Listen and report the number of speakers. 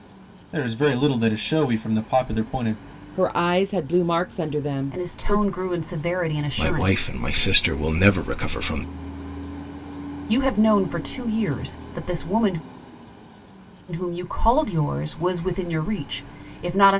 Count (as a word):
four